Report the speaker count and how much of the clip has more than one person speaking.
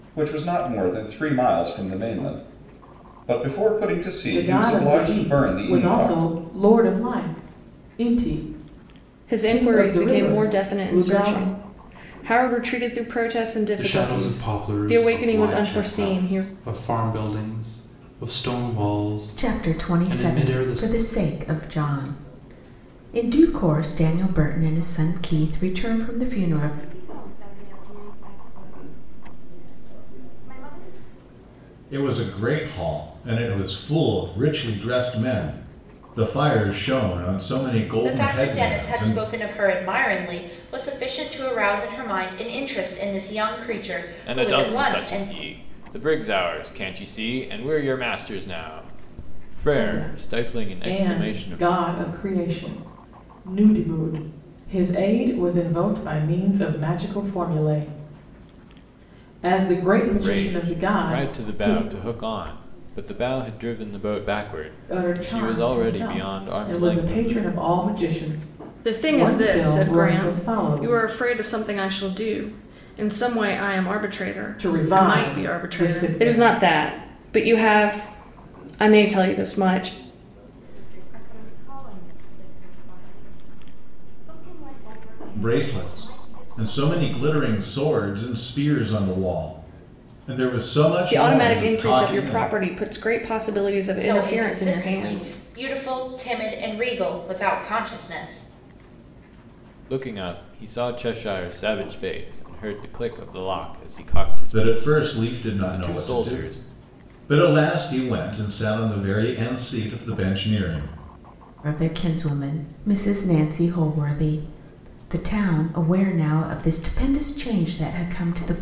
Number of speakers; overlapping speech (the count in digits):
9, about 27%